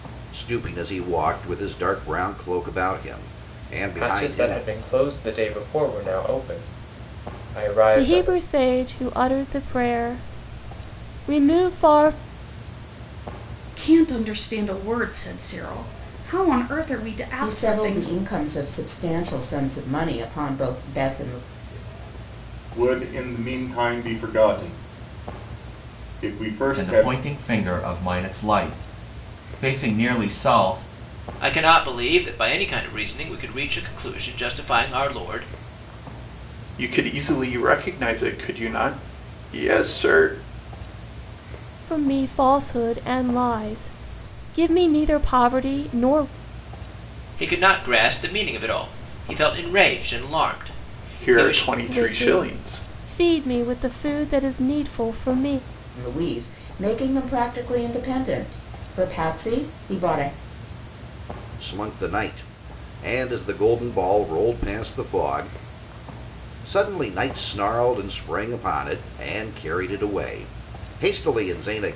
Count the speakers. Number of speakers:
9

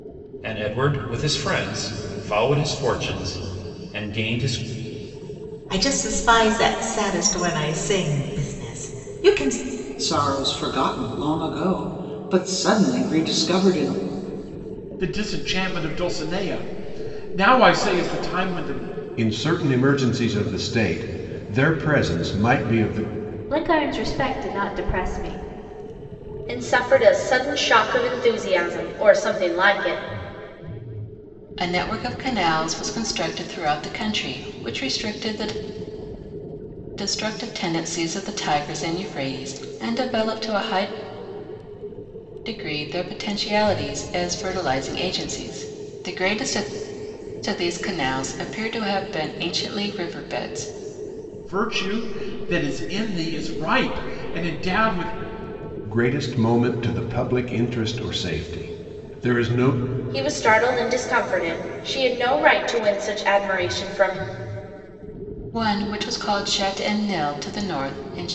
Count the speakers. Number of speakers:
8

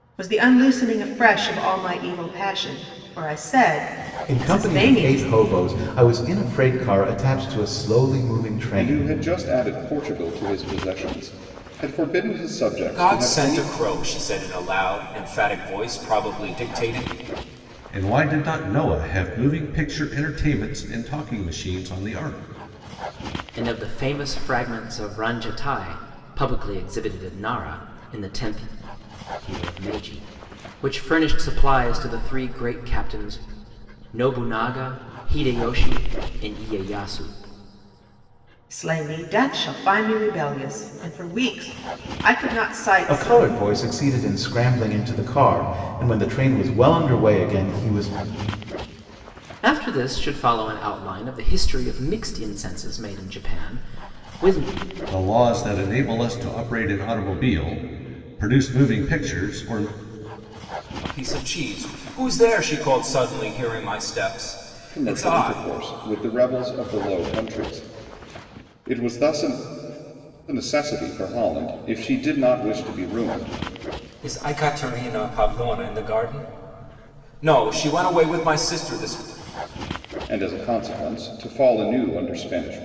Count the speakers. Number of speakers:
6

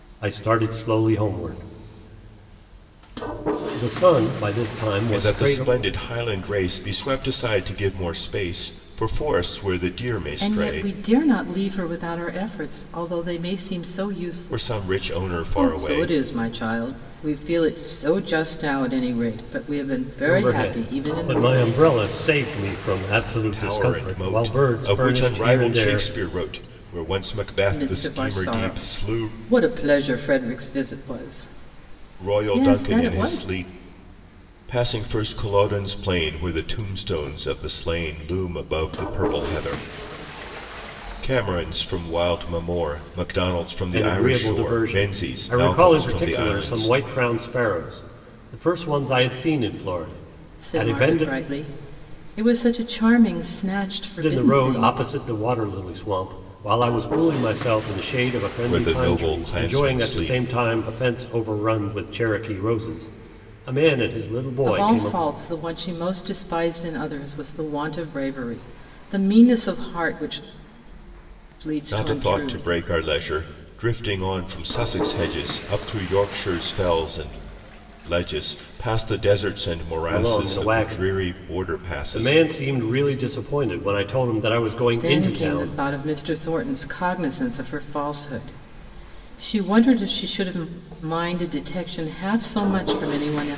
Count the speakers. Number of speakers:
3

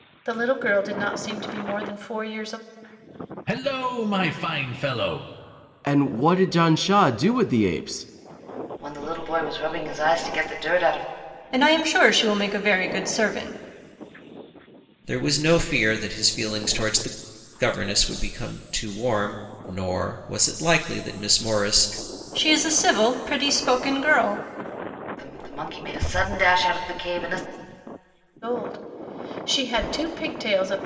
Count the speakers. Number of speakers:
6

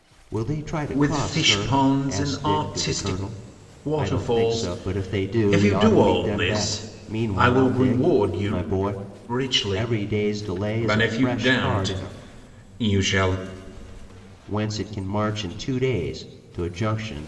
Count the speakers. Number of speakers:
2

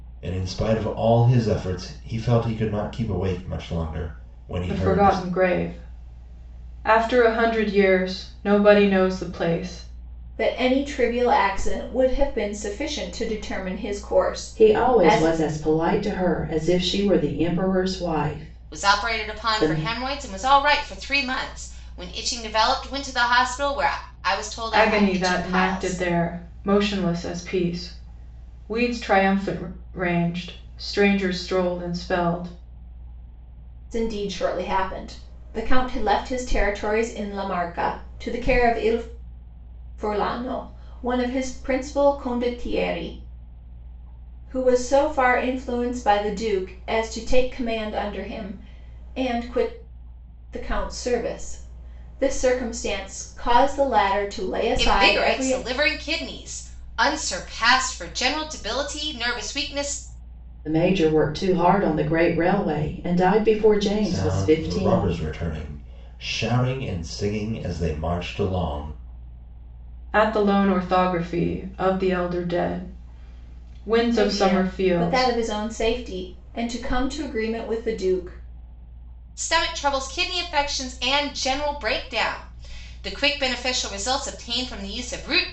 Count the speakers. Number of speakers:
5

